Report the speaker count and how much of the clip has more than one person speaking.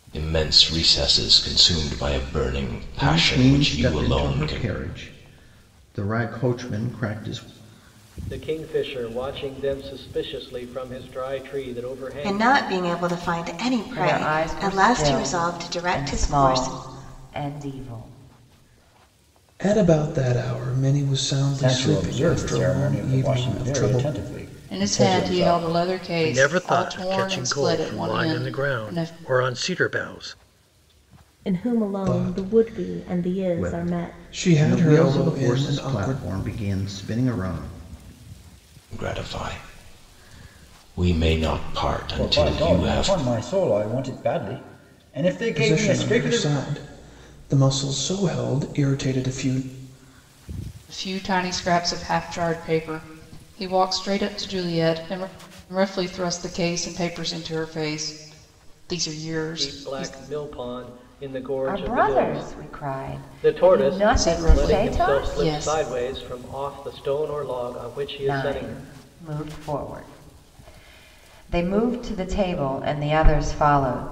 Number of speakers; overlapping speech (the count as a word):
ten, about 32%